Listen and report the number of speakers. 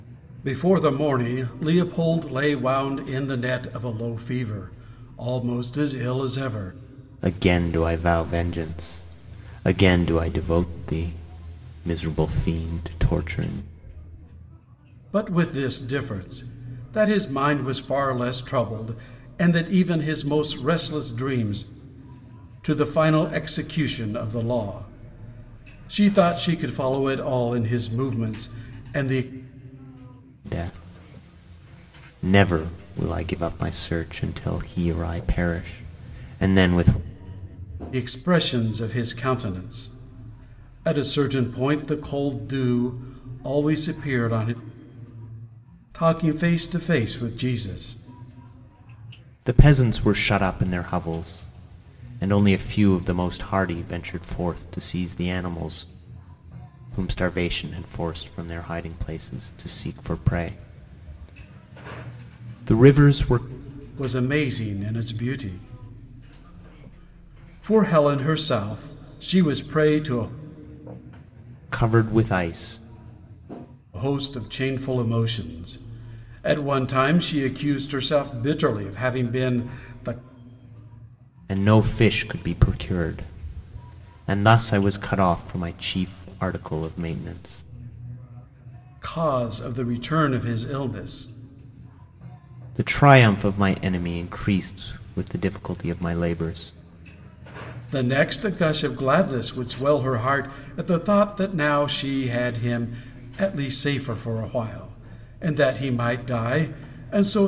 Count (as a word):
two